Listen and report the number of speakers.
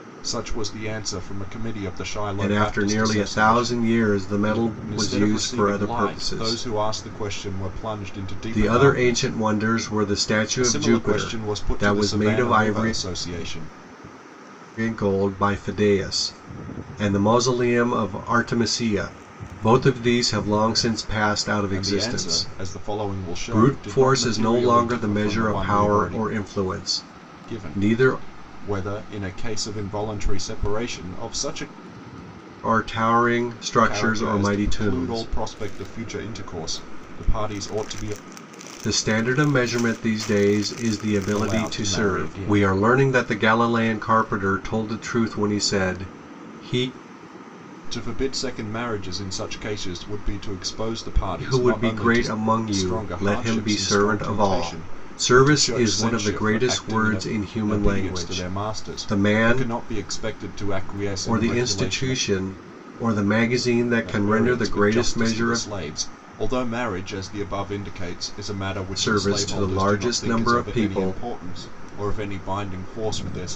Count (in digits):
2